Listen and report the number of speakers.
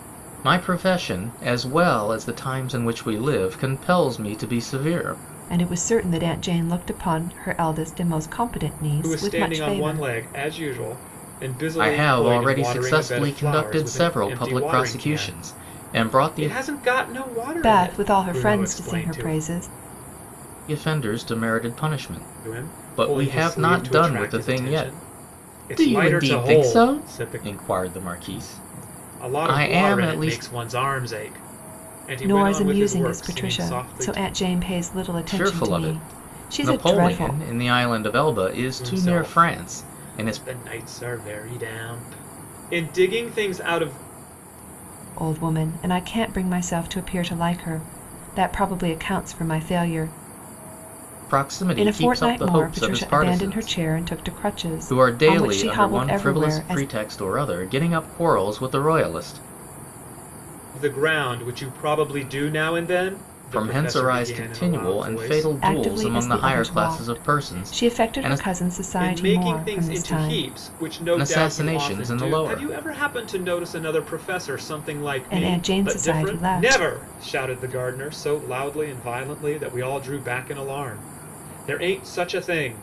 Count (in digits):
3